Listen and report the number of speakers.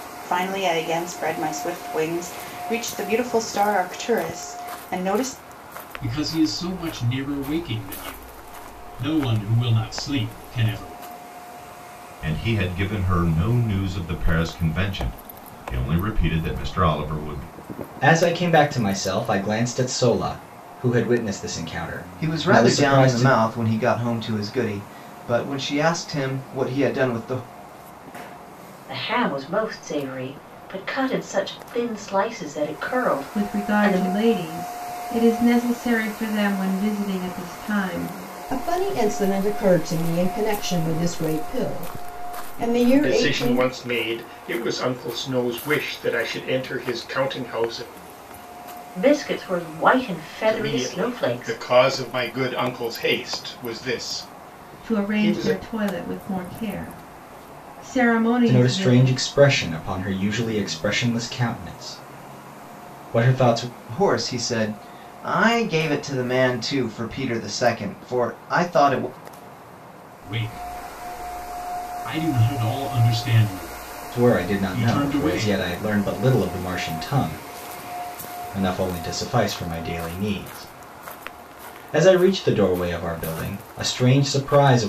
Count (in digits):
9